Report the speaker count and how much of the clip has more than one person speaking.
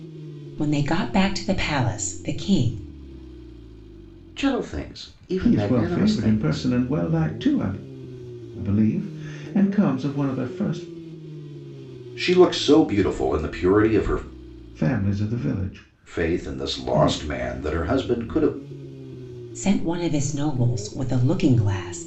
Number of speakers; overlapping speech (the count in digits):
3, about 11%